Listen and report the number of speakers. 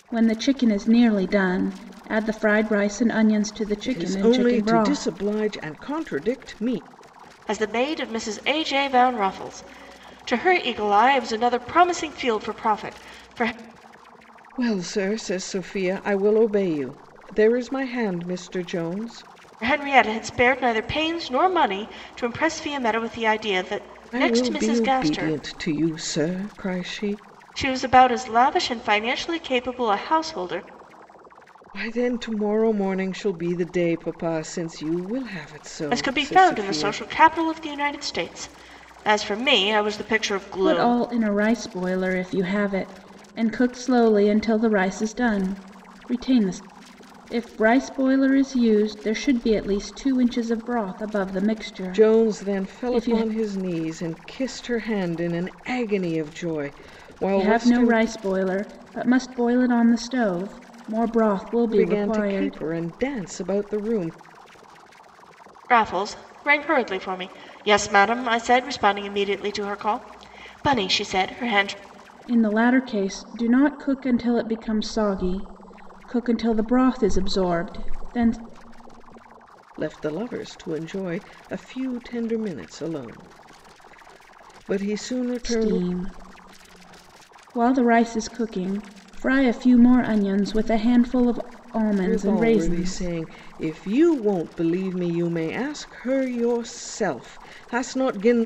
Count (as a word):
three